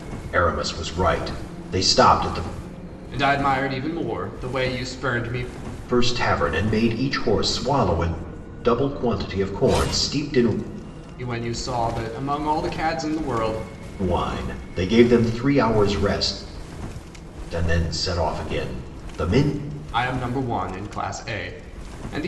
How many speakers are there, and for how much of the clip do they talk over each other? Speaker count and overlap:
two, no overlap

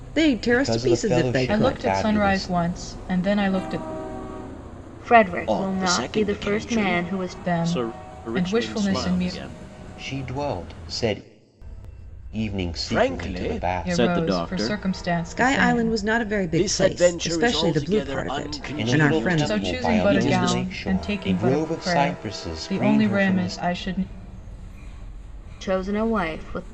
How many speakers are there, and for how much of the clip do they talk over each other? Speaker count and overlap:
five, about 59%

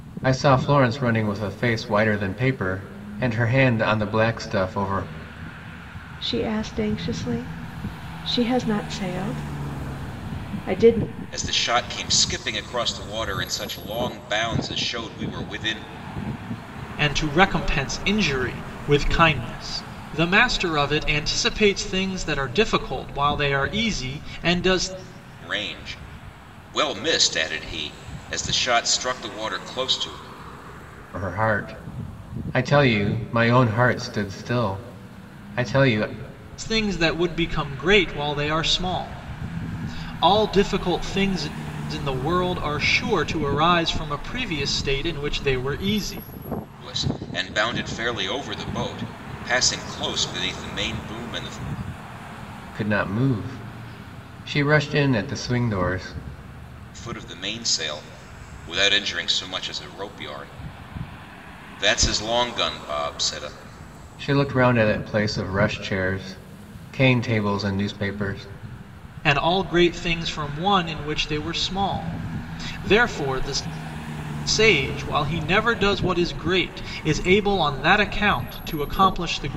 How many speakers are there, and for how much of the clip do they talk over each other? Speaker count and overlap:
four, no overlap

